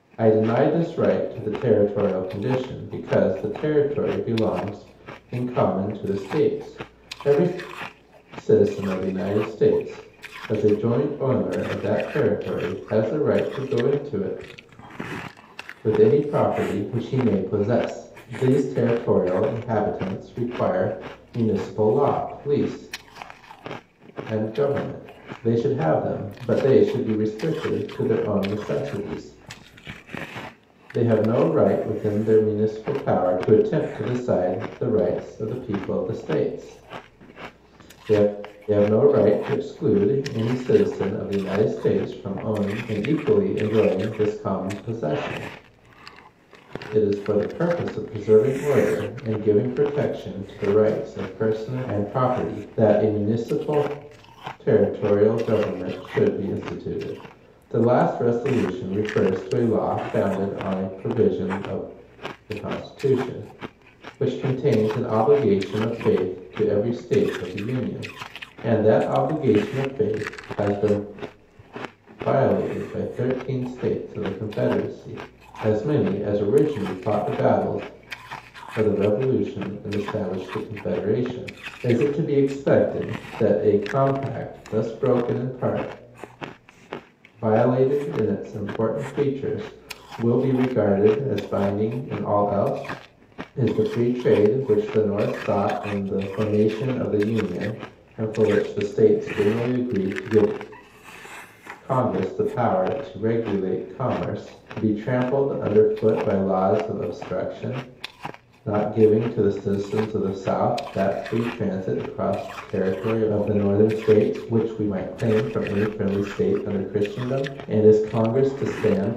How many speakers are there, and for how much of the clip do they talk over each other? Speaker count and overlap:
1, no overlap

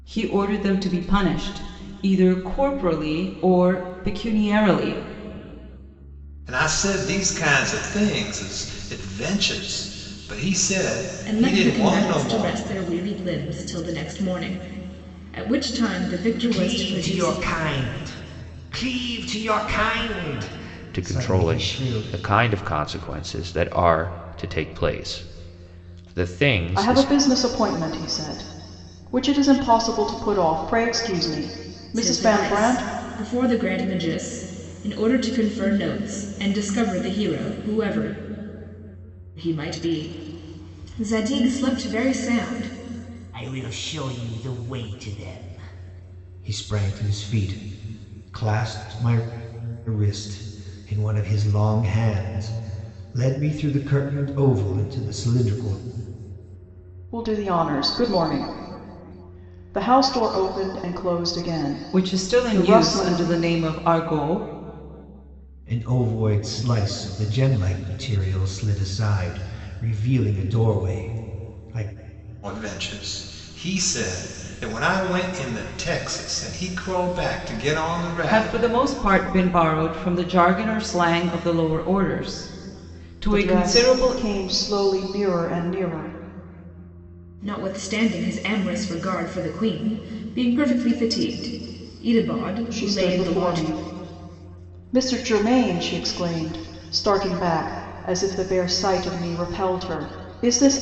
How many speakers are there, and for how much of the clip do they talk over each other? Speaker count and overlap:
6, about 9%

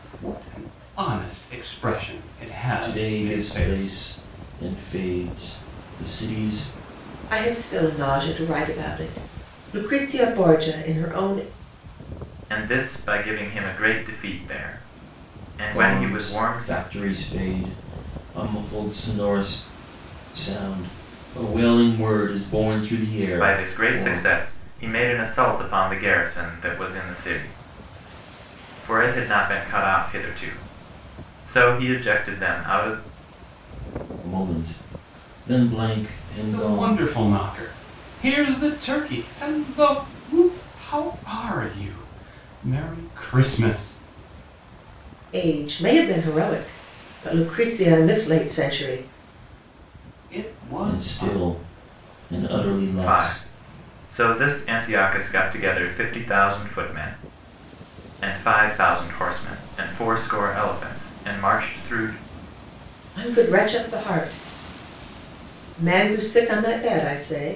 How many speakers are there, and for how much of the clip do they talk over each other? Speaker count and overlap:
4, about 7%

